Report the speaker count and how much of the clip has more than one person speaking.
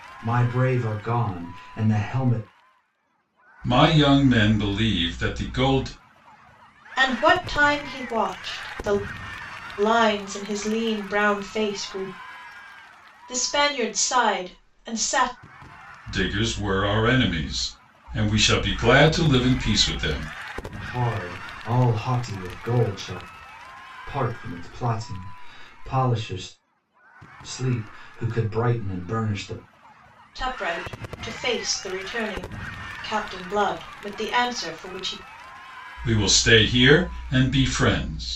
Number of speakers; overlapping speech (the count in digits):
3, no overlap